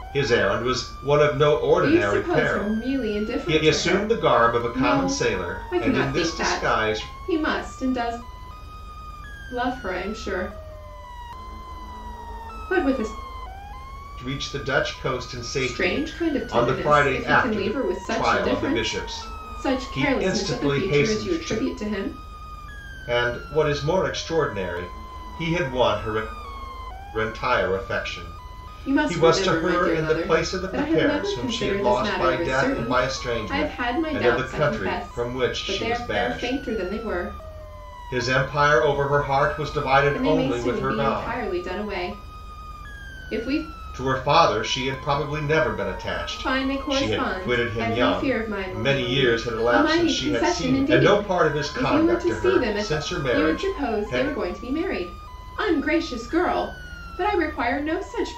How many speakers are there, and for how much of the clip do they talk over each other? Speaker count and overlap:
two, about 46%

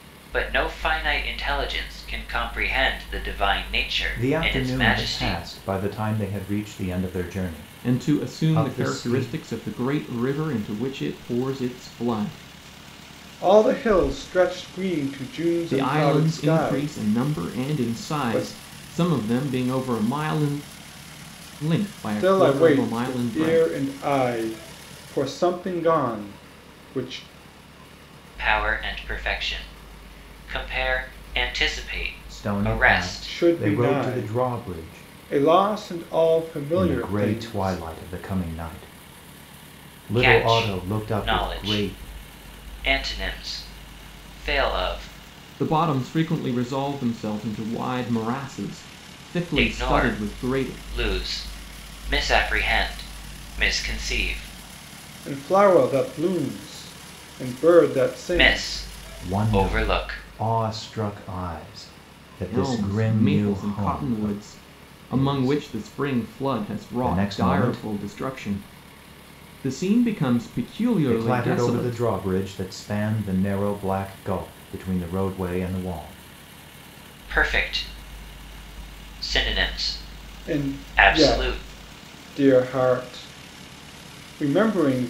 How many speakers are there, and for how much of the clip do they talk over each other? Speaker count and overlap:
four, about 27%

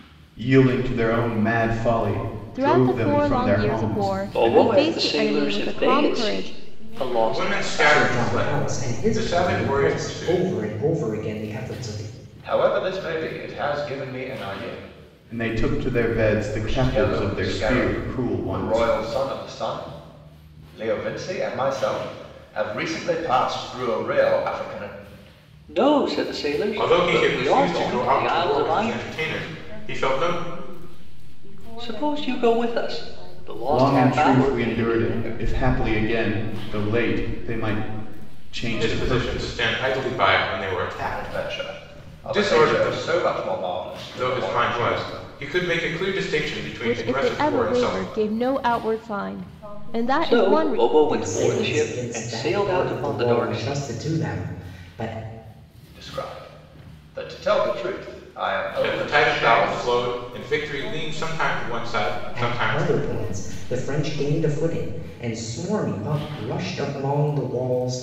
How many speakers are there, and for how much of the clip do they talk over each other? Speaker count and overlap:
seven, about 51%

